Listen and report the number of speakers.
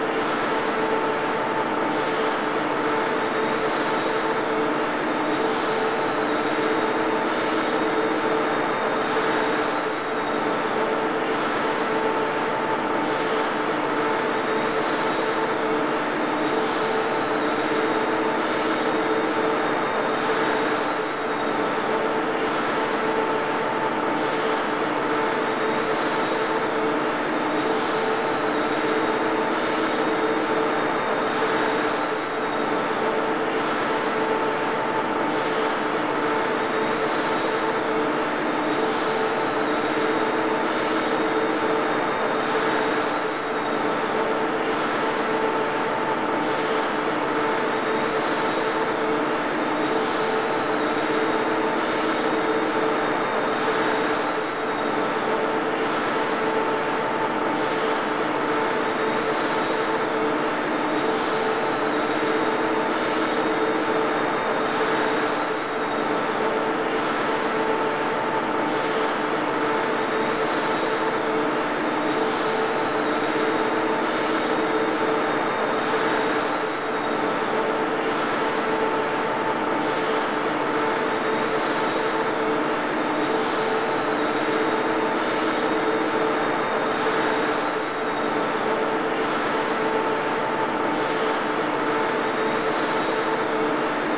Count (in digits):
0